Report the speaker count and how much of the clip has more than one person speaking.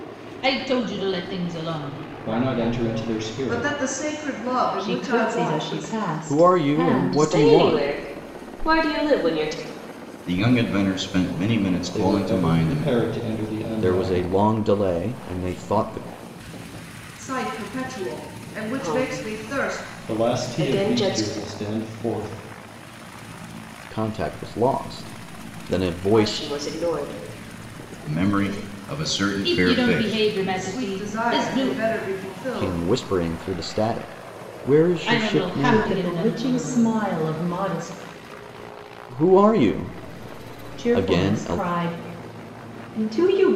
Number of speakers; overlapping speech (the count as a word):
seven, about 34%